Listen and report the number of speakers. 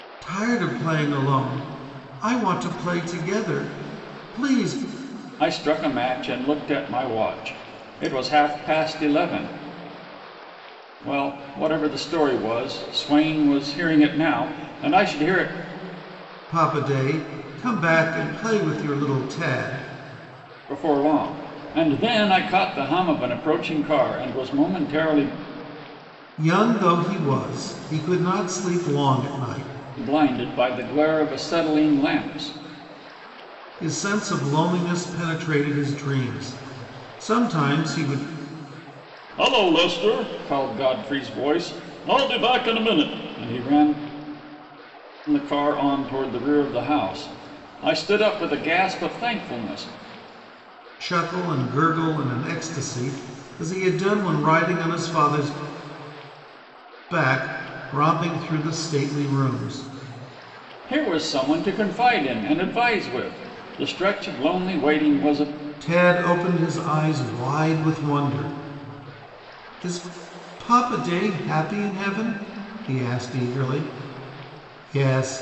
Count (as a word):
two